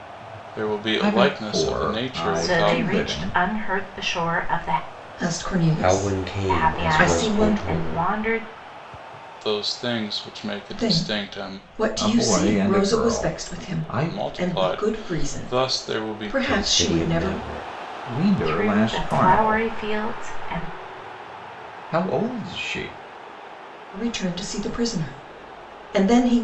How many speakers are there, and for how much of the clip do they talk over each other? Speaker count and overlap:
5, about 47%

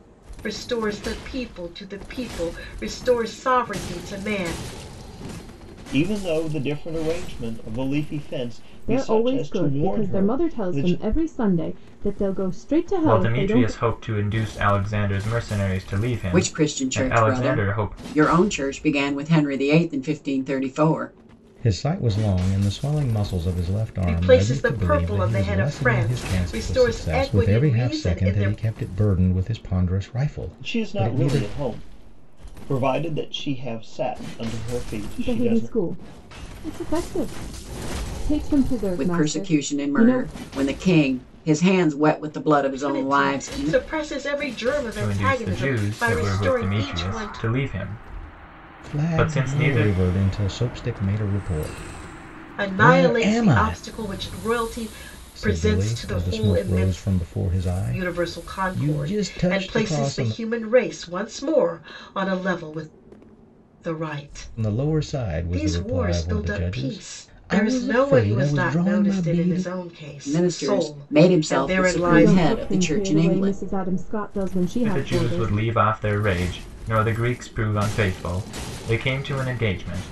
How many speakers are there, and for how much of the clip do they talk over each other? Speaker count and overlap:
6, about 39%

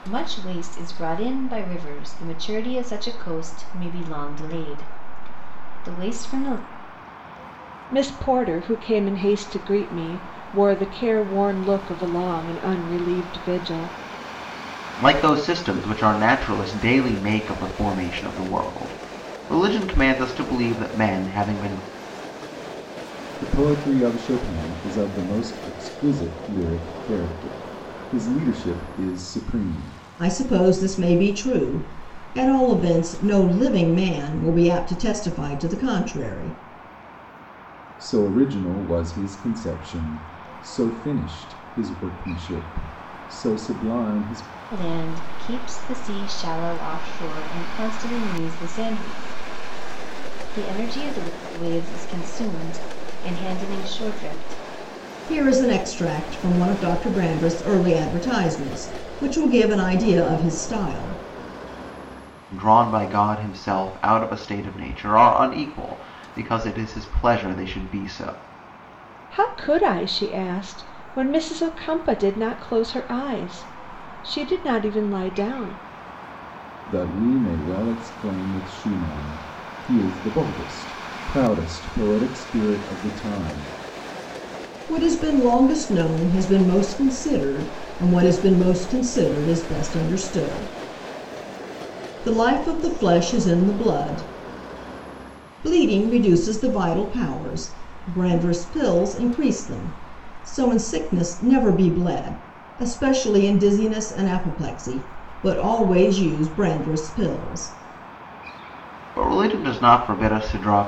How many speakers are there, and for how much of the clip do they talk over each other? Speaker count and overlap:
5, no overlap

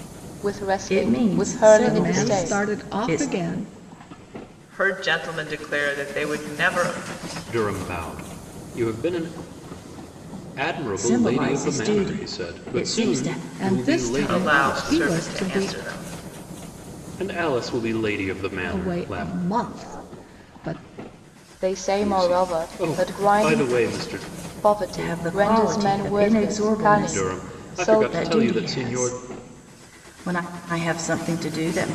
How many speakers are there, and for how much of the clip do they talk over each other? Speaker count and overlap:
5, about 43%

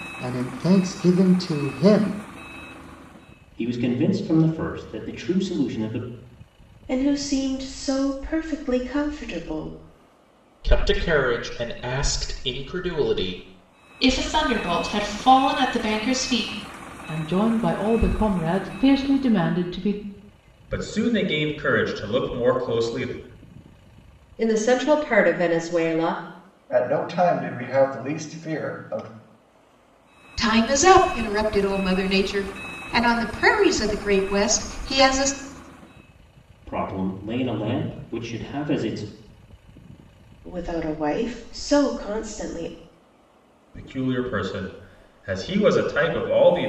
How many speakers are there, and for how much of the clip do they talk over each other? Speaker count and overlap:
10, no overlap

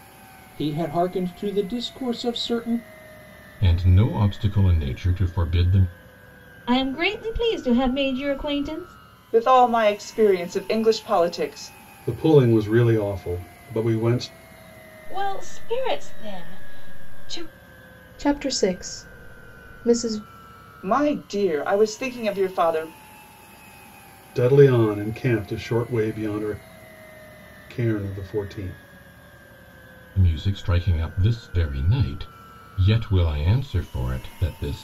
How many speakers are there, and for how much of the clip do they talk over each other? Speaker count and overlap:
7, no overlap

